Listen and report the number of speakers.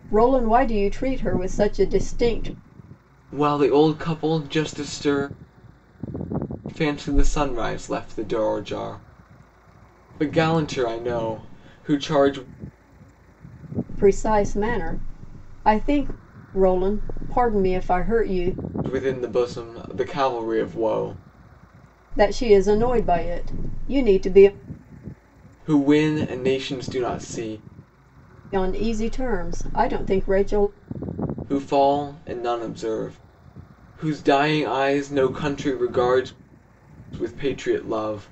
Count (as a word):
two